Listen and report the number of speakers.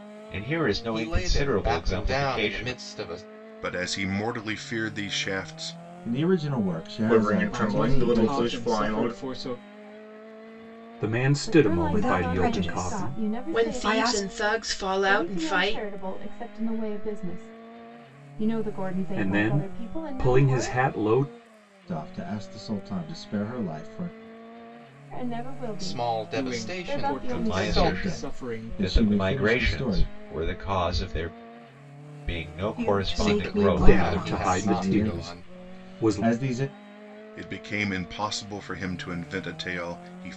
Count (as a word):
ten